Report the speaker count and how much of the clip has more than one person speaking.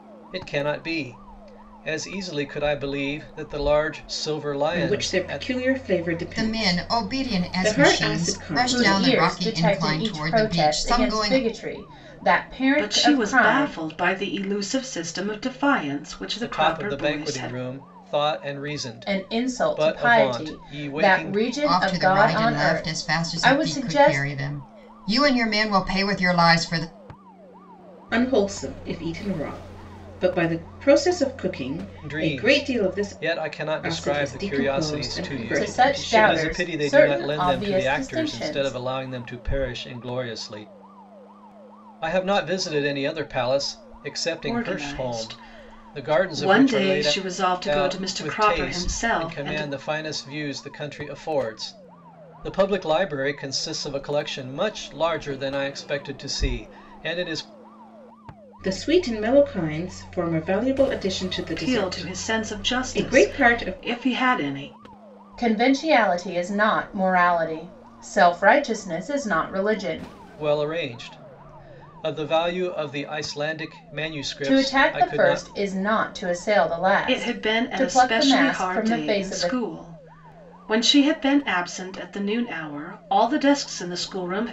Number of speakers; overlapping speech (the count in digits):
5, about 36%